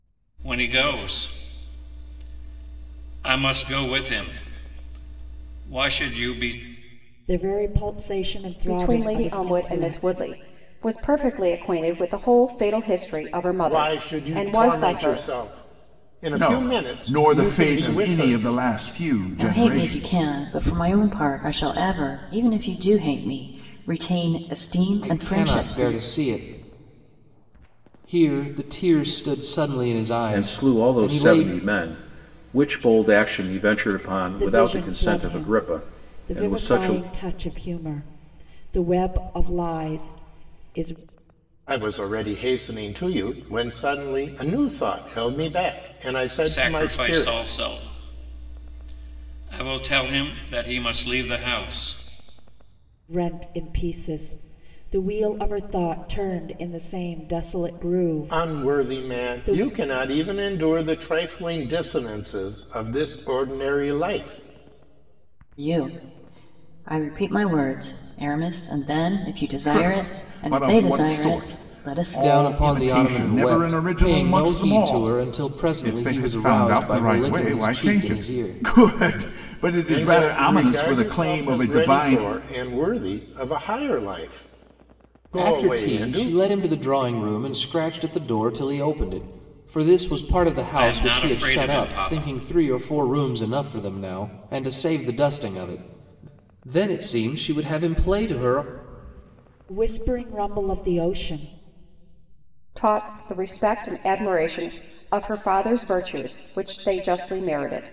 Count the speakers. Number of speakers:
8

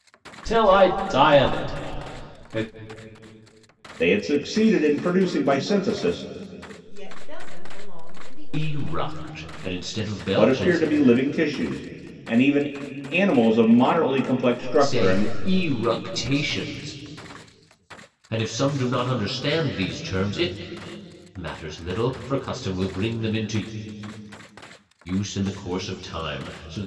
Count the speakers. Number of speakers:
4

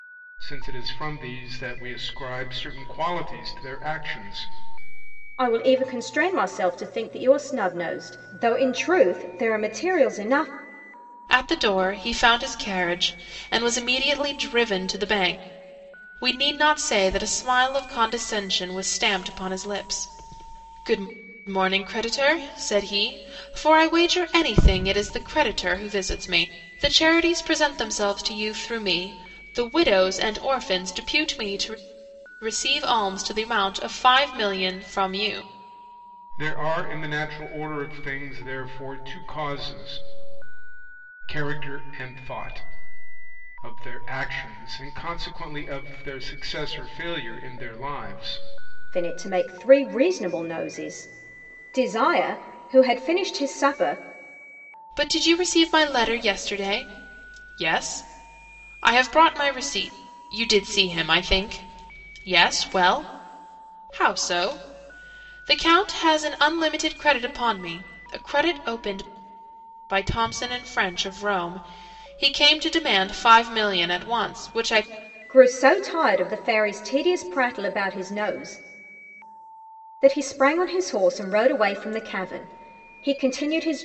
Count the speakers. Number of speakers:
3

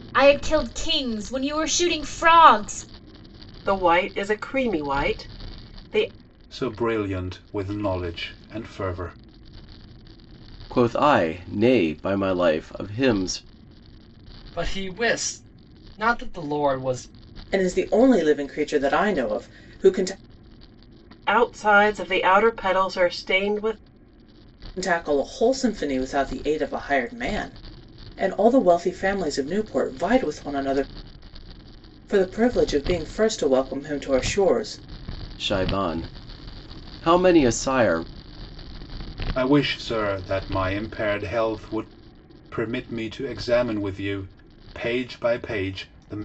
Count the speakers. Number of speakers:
6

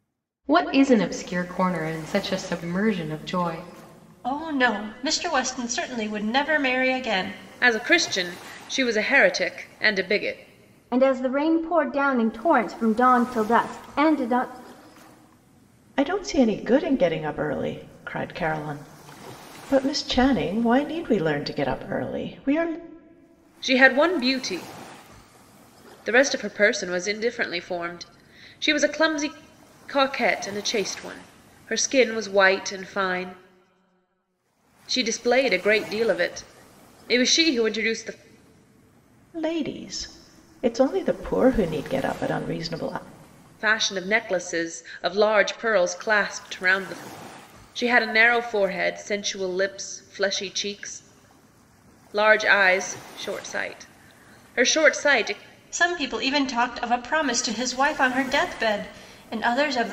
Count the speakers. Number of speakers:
5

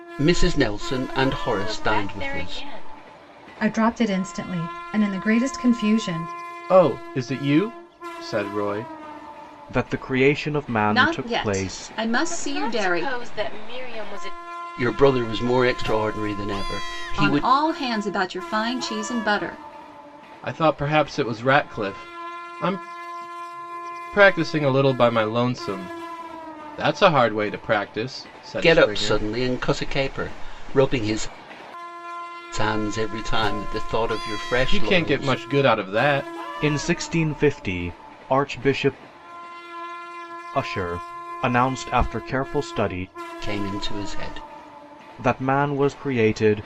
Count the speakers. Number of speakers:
6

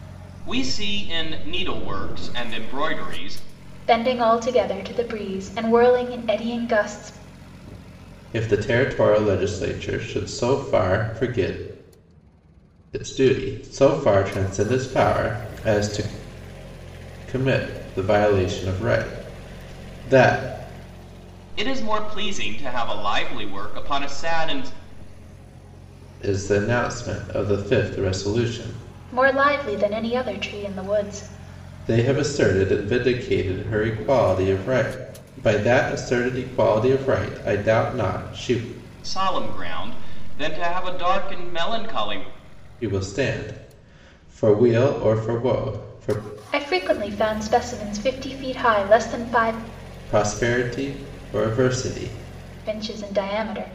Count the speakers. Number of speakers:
3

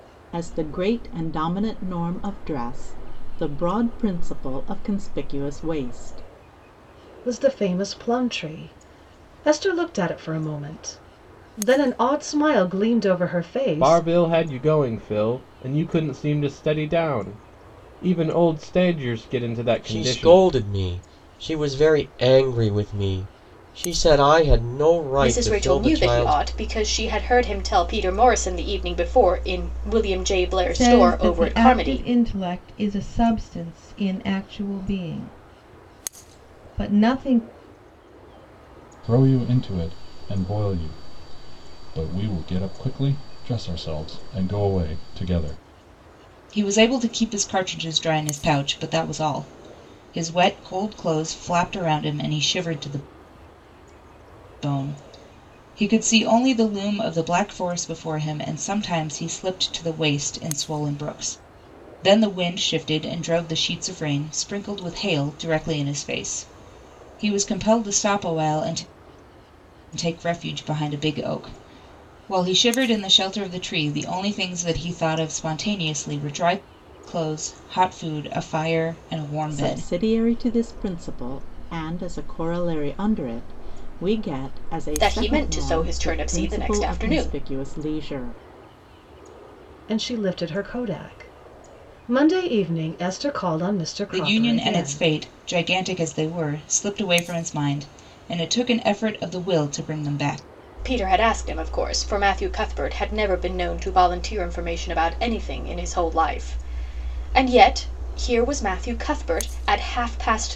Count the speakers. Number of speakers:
8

